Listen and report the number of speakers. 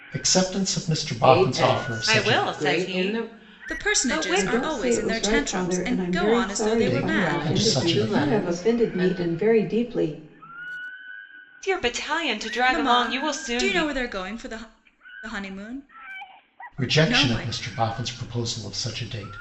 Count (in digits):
5